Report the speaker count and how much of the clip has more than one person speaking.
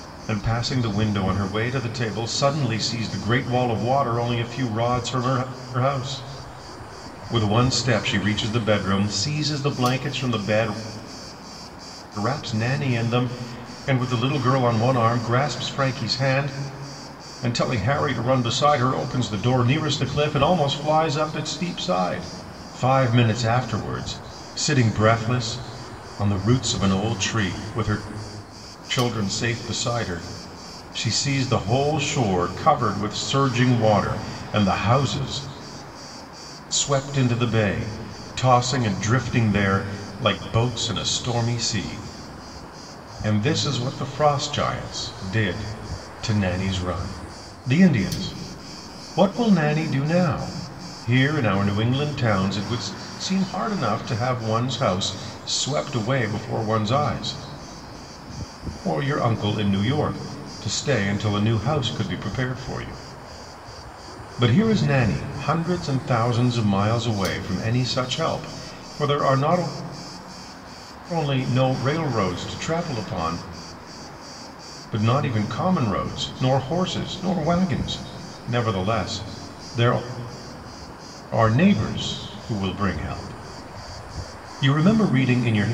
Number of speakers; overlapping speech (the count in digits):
1, no overlap